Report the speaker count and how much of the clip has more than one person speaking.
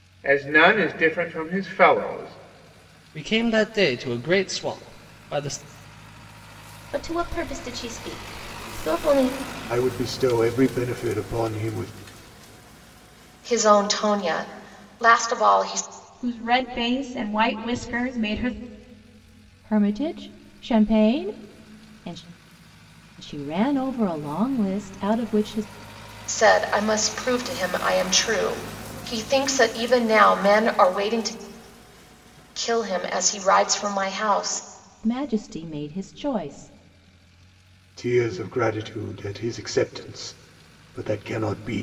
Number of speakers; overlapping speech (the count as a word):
seven, no overlap